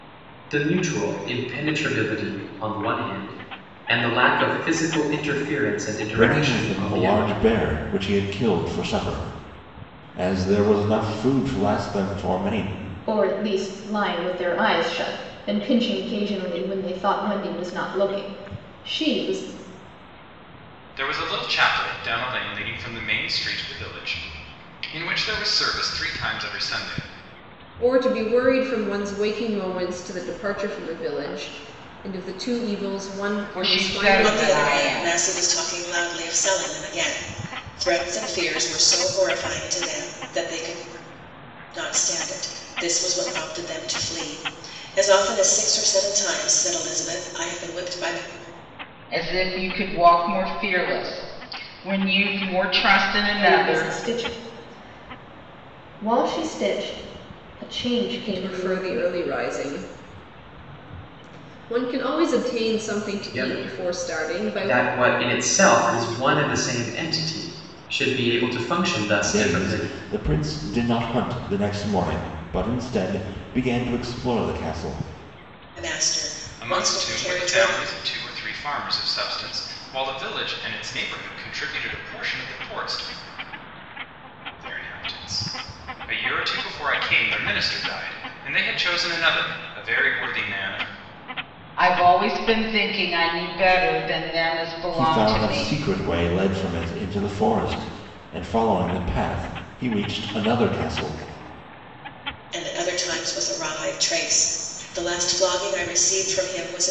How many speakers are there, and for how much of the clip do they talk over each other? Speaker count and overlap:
7, about 8%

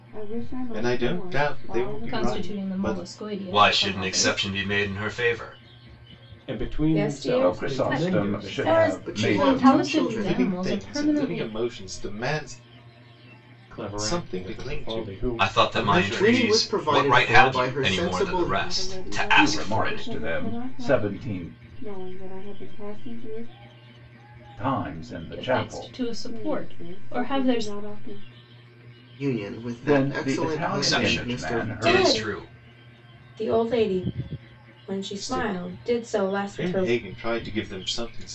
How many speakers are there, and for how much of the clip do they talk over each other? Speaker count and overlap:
9, about 57%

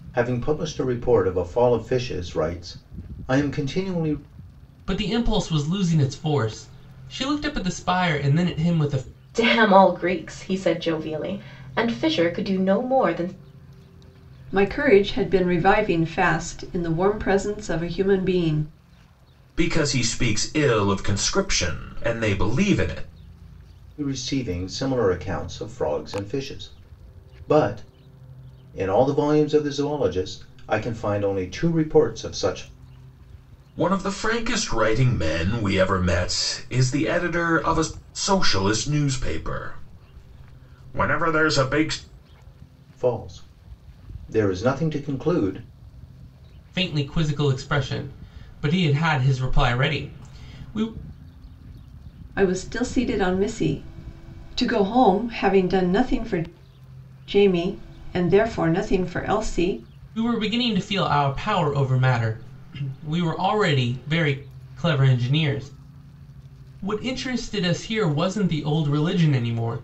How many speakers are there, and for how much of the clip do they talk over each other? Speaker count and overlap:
5, no overlap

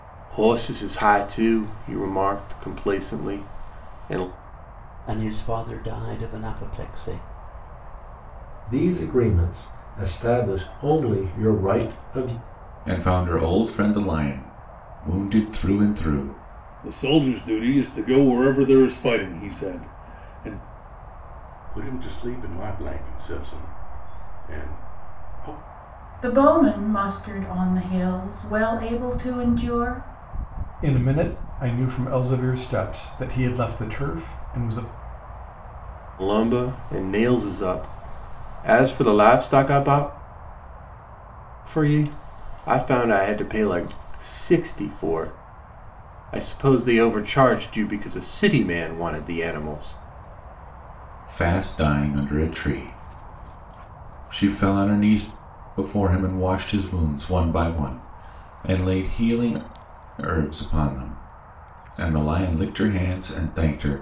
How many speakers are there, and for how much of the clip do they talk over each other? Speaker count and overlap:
8, no overlap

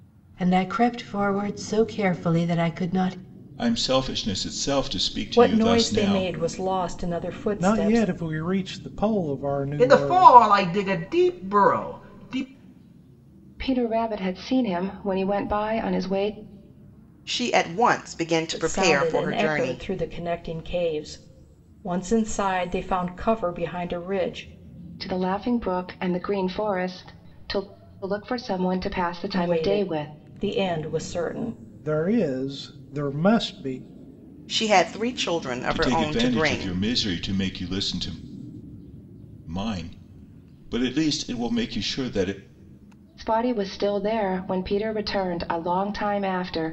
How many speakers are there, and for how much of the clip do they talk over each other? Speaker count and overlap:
7, about 12%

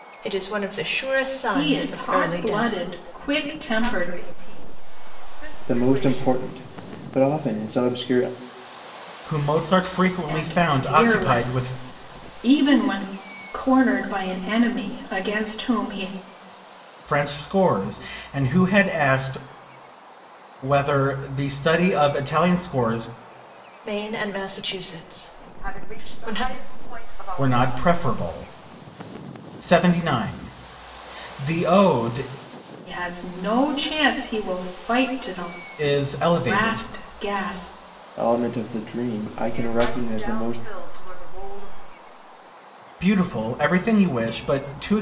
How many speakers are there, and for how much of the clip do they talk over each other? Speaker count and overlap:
5, about 18%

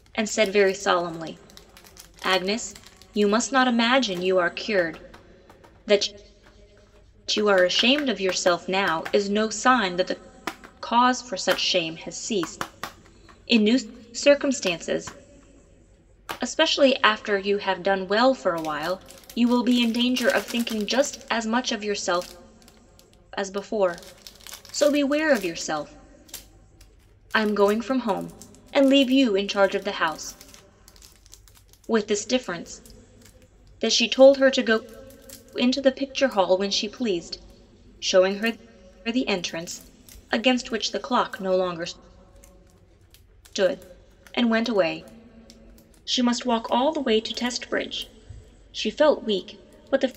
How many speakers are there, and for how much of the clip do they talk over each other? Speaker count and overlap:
1, no overlap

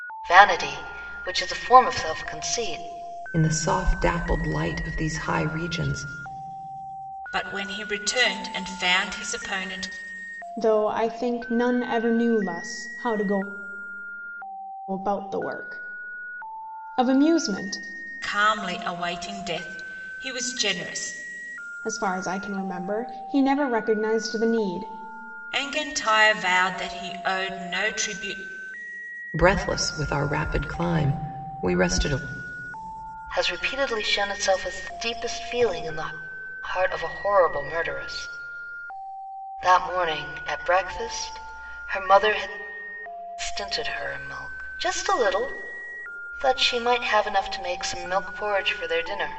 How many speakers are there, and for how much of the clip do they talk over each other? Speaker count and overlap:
4, no overlap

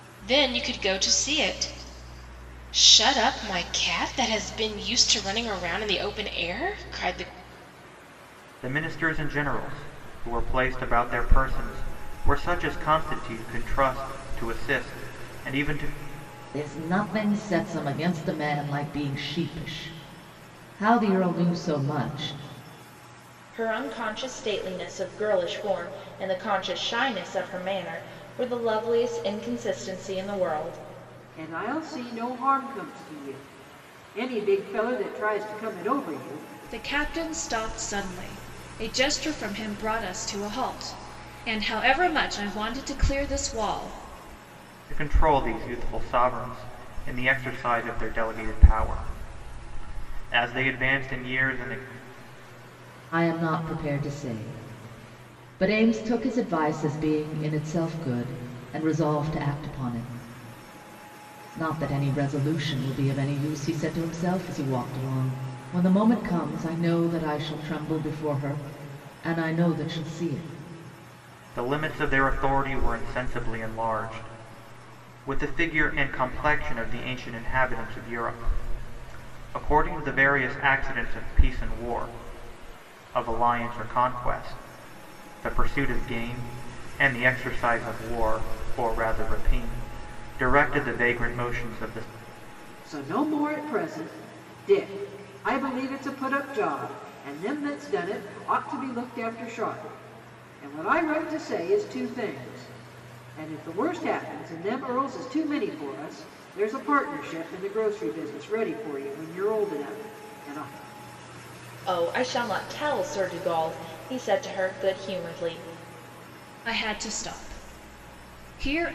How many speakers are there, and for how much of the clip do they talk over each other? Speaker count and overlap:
6, no overlap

